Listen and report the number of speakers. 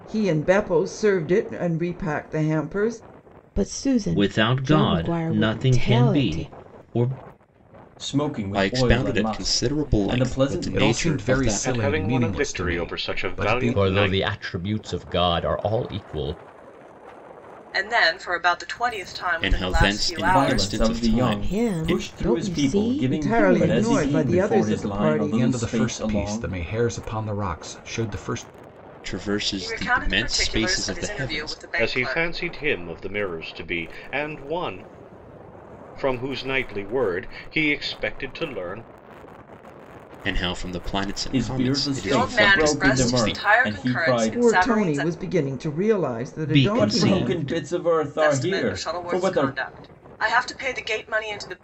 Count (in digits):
9